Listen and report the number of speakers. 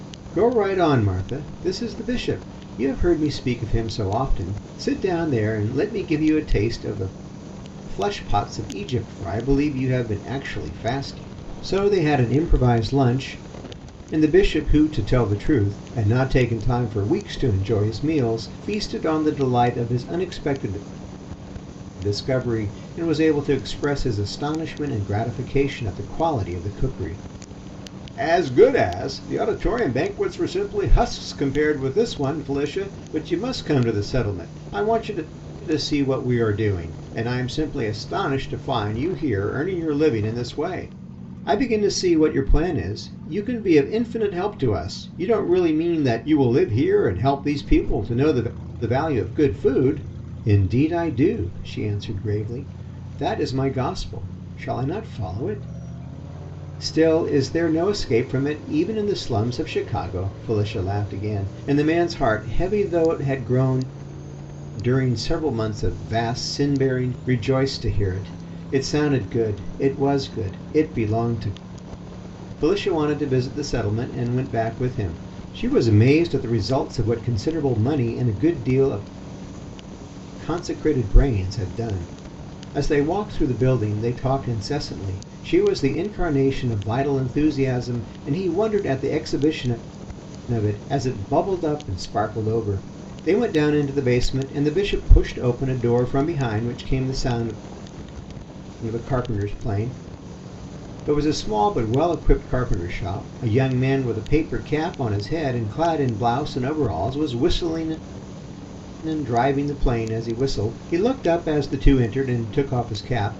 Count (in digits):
1